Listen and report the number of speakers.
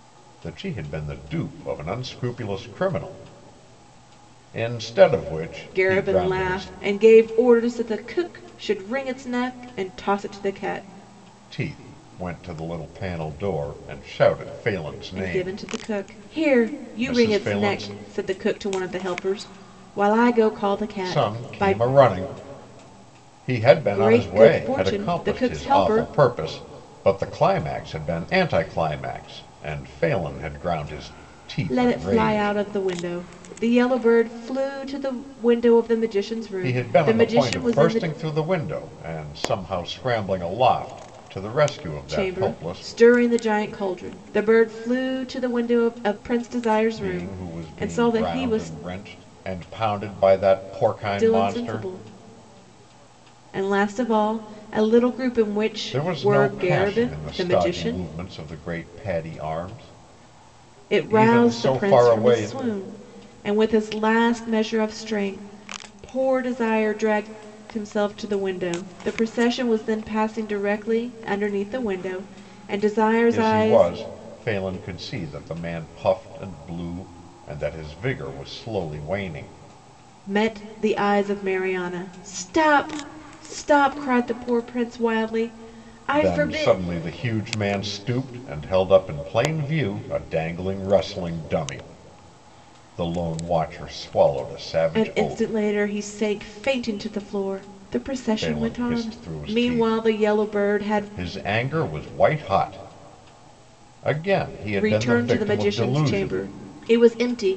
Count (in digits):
2